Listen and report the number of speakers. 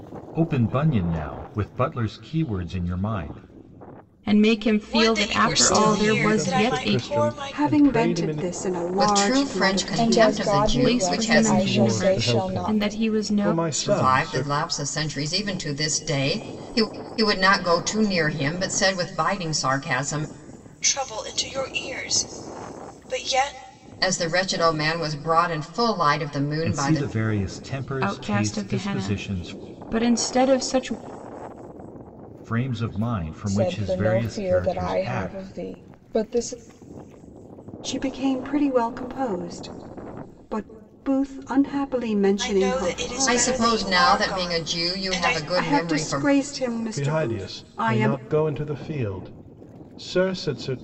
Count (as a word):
seven